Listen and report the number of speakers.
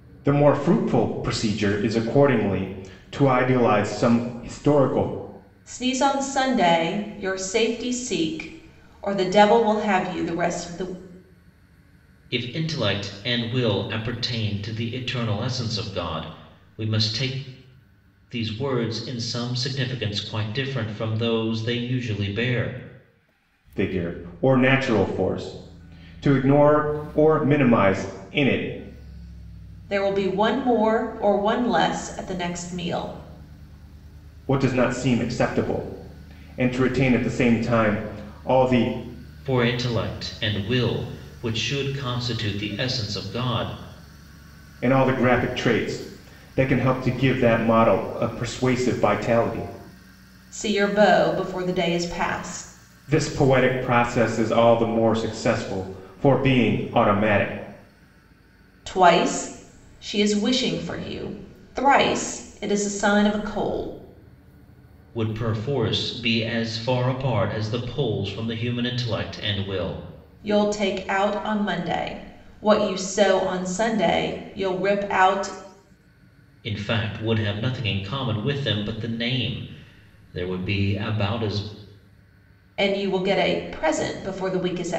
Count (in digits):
3